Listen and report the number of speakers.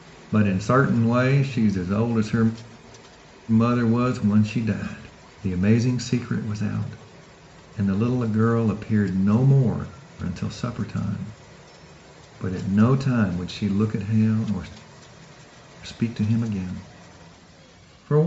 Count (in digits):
1